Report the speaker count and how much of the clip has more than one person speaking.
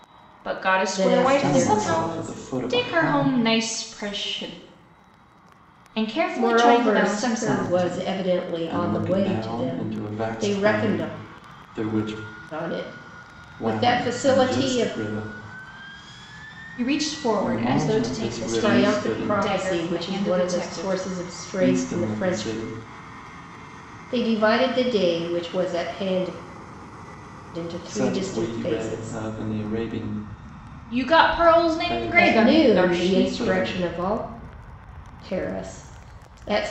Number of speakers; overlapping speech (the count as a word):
three, about 44%